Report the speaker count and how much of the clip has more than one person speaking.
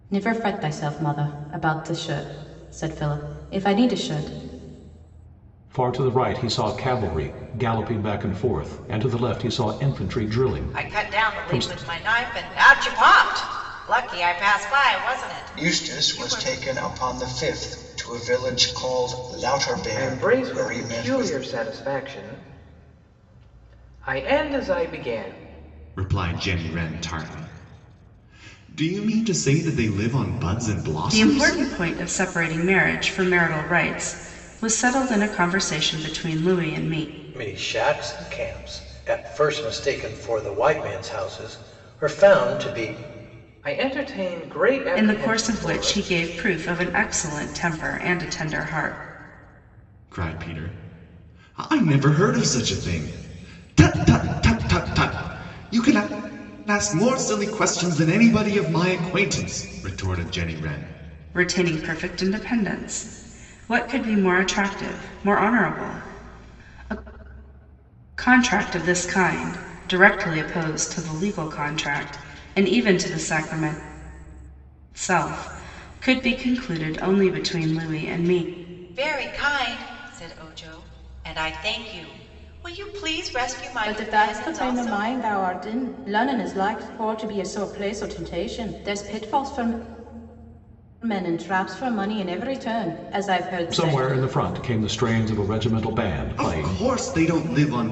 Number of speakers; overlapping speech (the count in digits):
8, about 7%